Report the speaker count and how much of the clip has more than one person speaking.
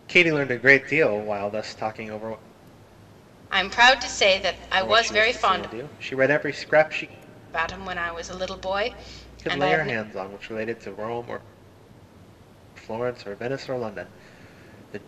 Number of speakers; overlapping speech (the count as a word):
two, about 11%